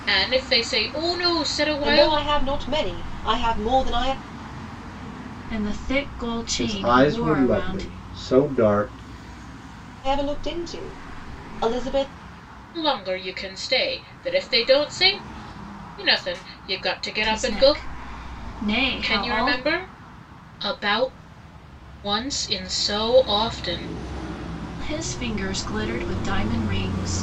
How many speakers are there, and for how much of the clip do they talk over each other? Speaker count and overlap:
4, about 11%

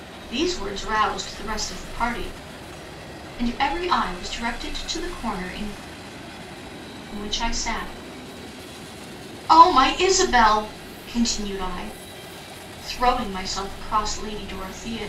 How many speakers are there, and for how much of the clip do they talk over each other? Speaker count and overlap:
1, no overlap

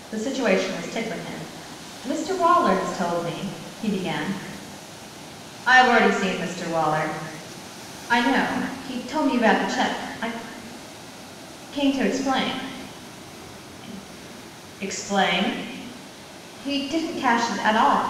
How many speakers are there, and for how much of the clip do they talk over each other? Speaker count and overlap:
1, no overlap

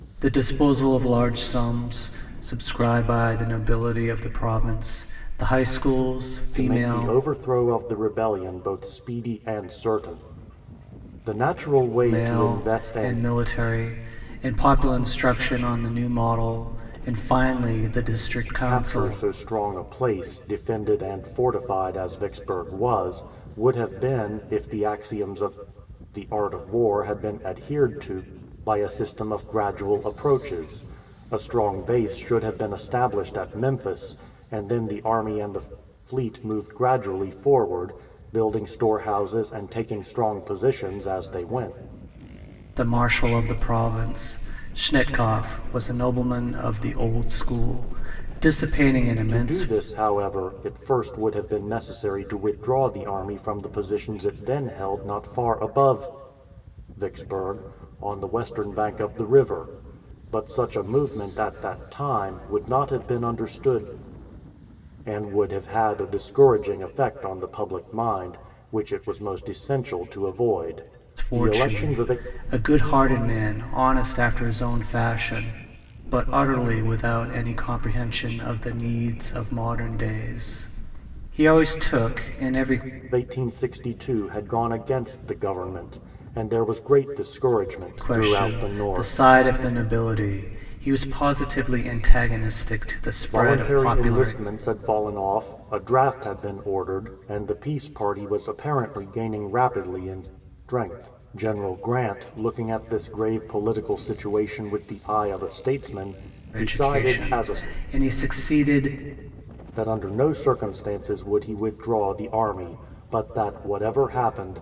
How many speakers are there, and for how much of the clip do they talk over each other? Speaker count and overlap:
2, about 7%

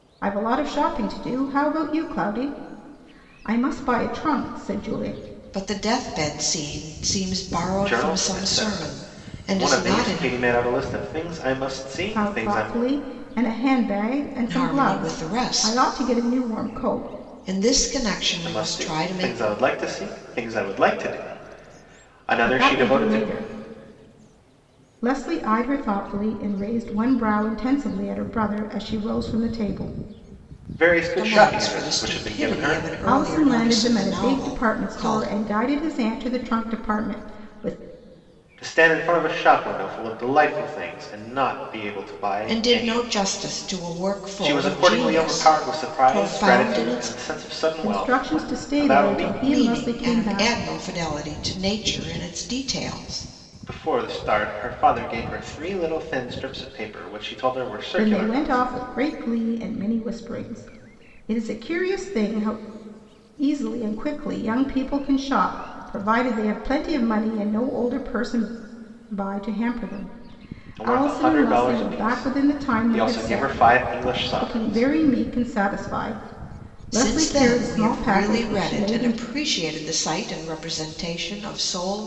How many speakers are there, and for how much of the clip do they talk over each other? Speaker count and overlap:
3, about 30%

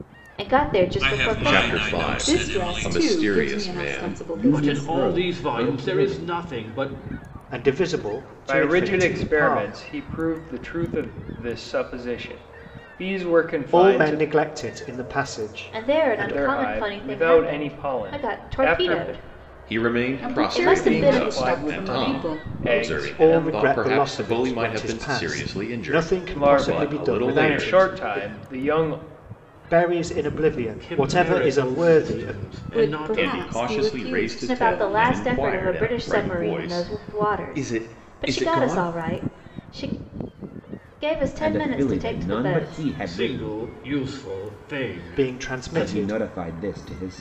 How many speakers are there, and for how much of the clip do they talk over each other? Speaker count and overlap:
8, about 64%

